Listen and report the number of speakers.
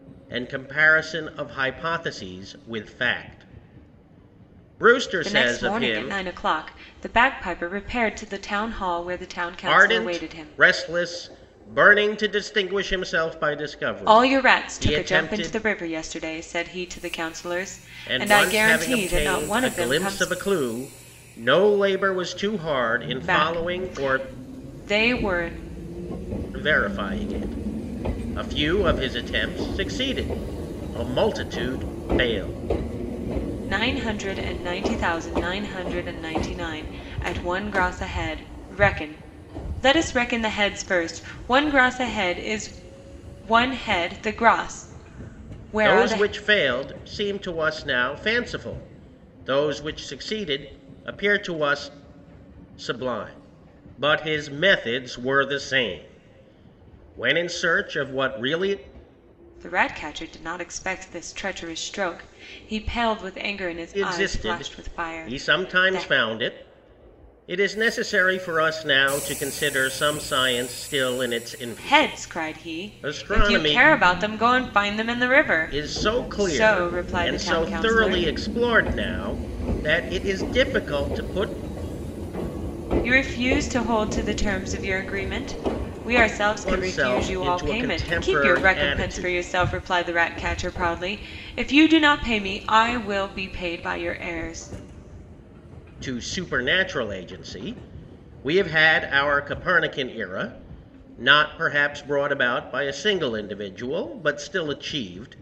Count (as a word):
two